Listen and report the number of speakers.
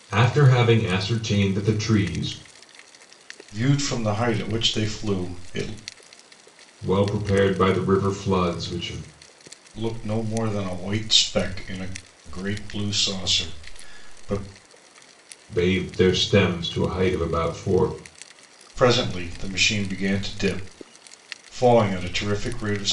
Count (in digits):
2